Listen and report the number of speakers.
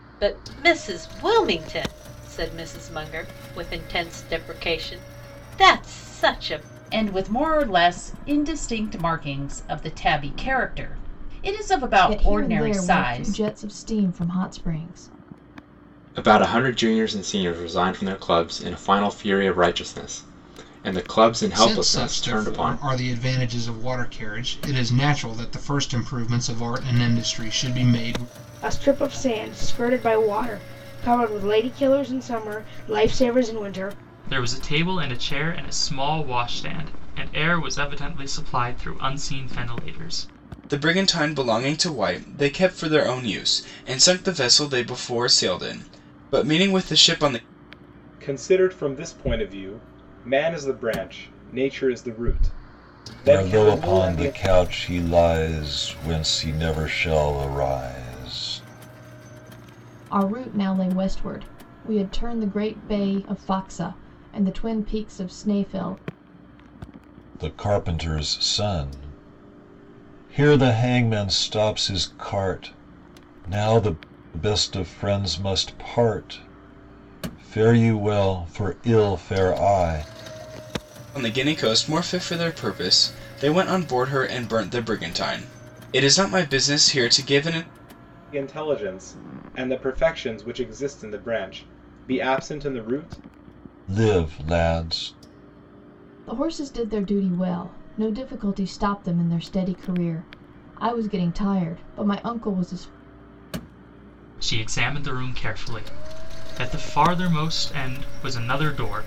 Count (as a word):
ten